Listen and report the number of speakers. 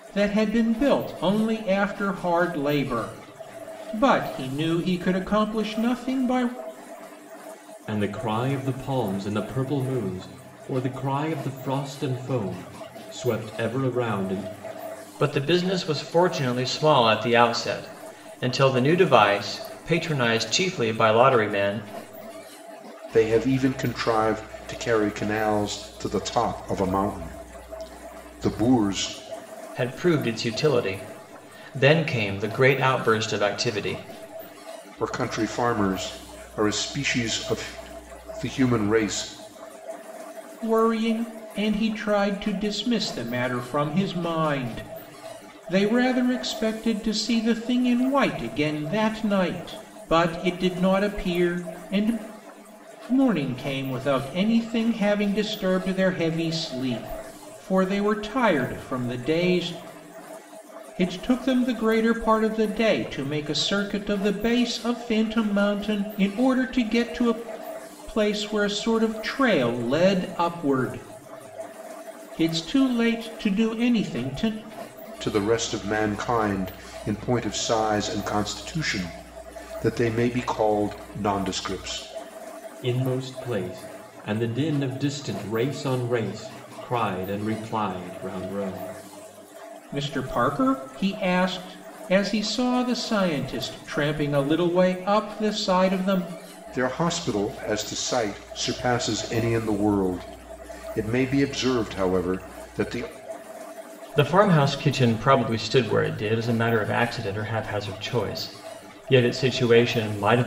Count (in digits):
4